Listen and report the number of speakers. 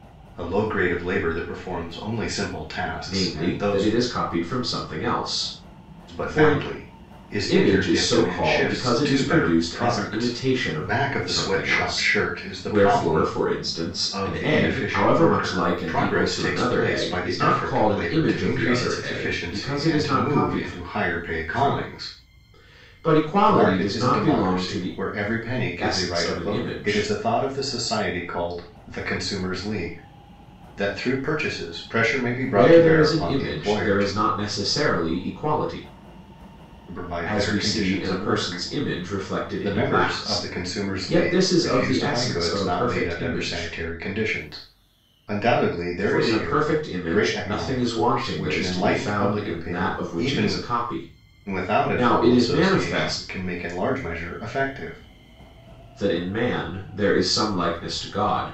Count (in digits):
2